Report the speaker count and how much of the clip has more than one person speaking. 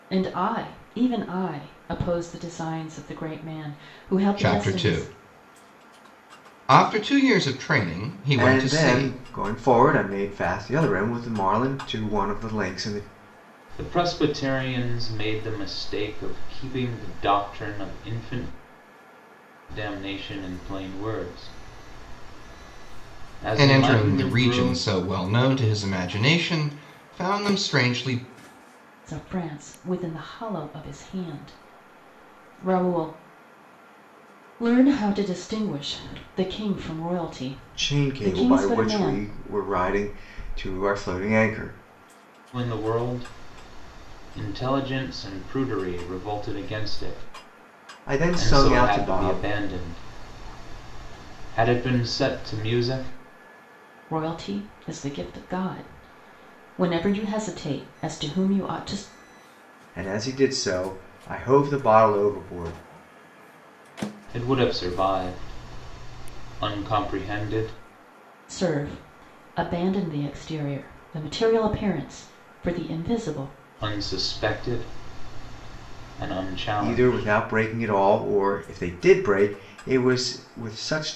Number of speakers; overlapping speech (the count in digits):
4, about 7%